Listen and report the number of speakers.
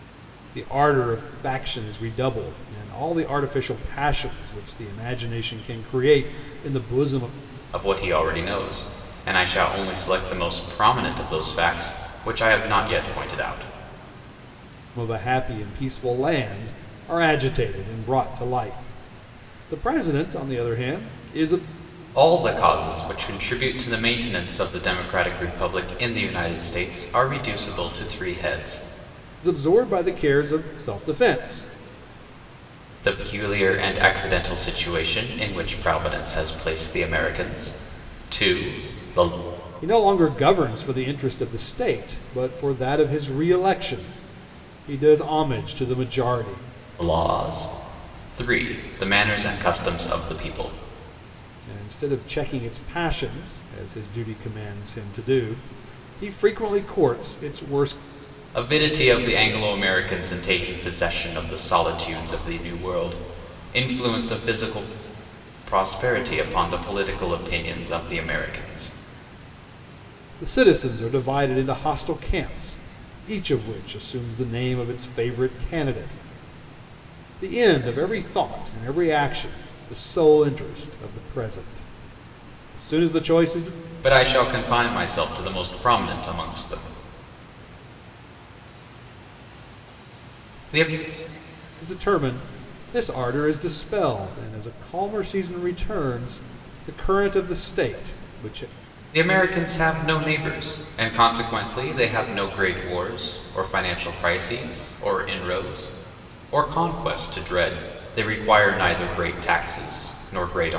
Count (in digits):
2